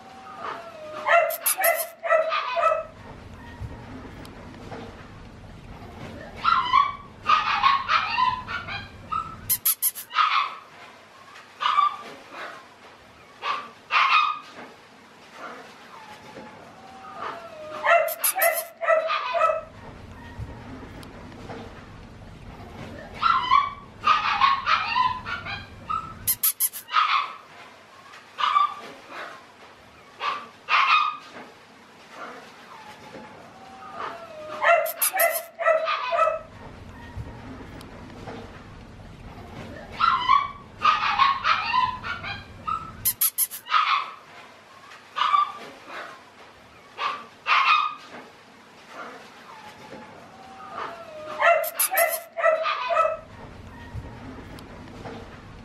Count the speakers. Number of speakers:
0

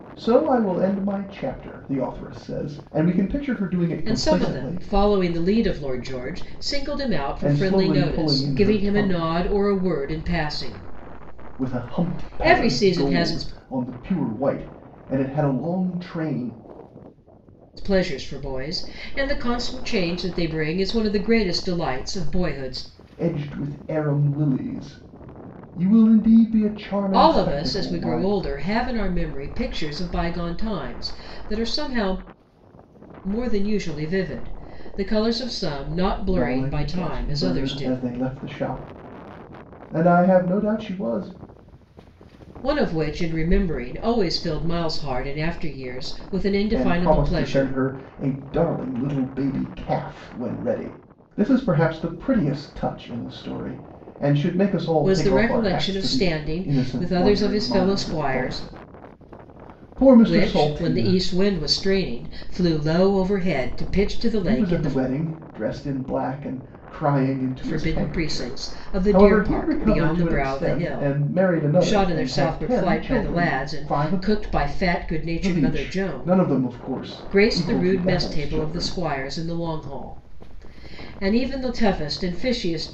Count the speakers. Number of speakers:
2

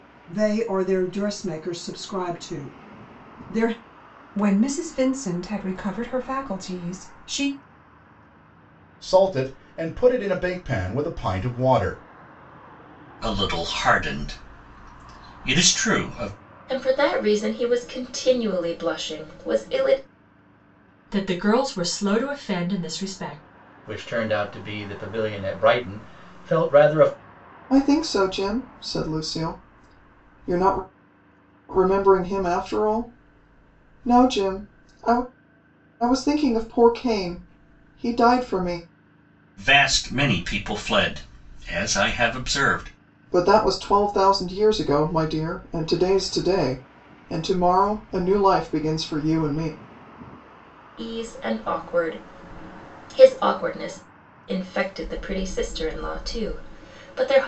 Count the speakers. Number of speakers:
8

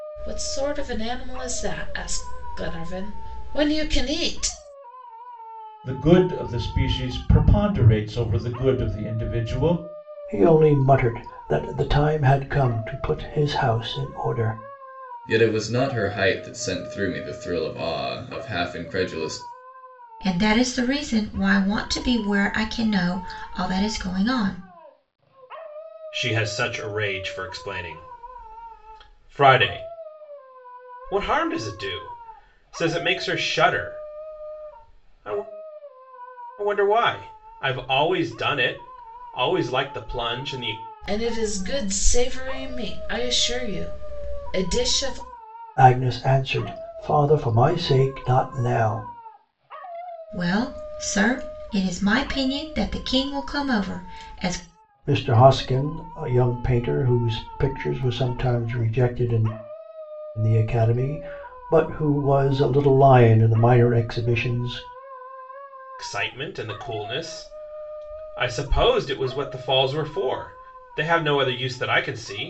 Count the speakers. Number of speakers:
6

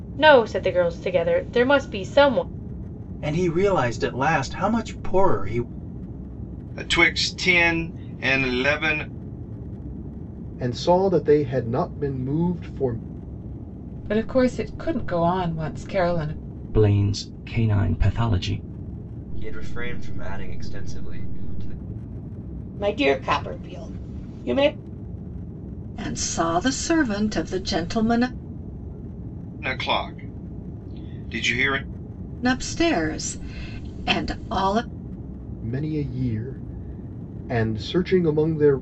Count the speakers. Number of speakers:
9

